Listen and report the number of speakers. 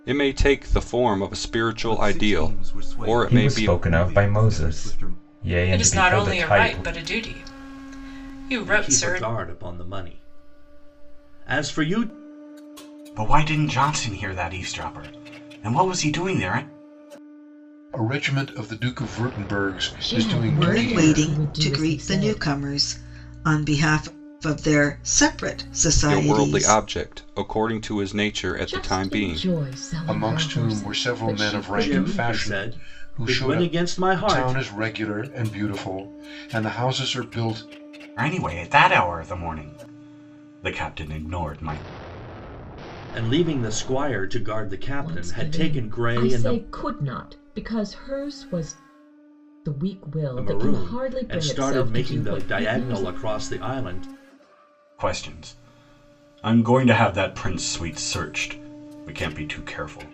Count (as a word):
nine